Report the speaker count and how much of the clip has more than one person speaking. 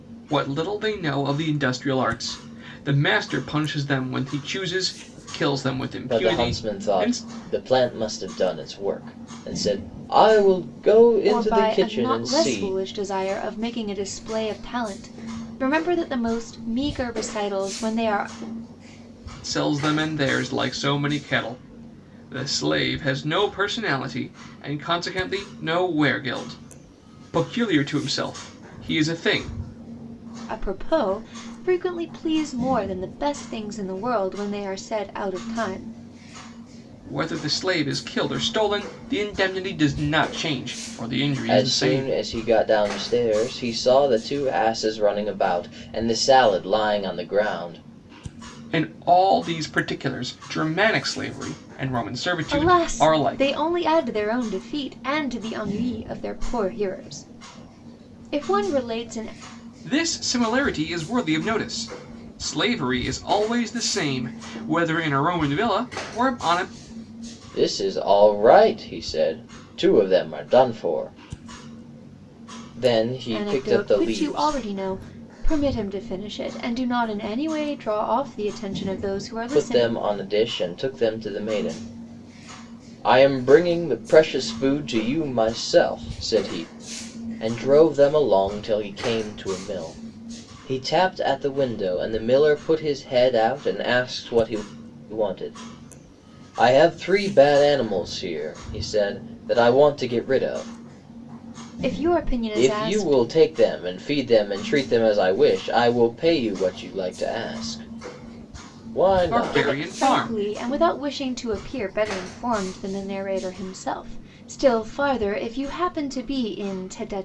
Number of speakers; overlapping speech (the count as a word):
three, about 7%